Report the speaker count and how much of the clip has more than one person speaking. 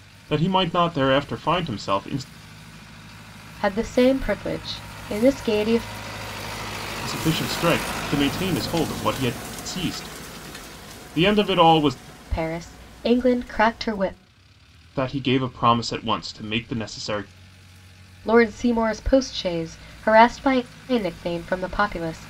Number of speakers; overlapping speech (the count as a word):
two, no overlap